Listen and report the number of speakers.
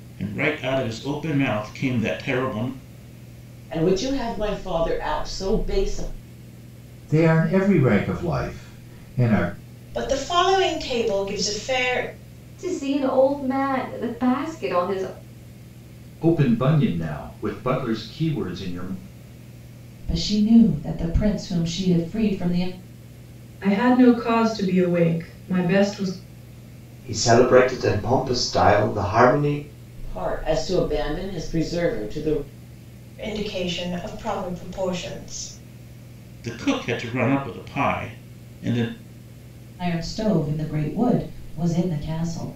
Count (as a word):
nine